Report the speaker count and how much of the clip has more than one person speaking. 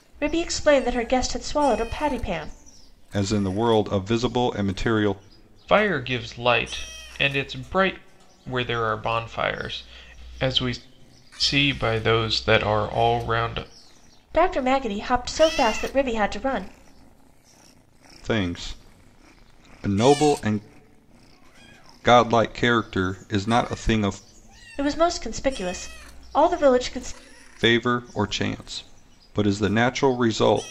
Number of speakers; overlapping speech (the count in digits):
3, no overlap